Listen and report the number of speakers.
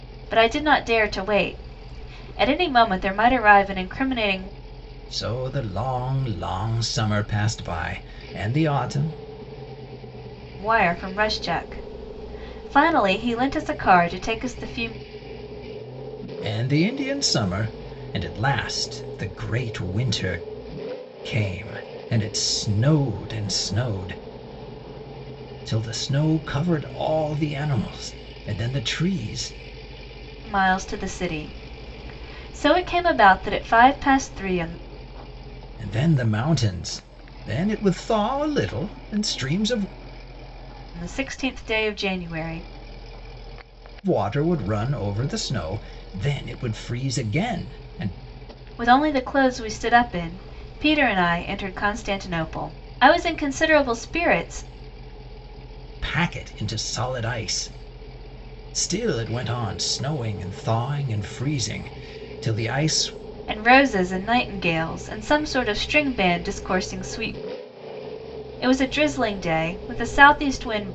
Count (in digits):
2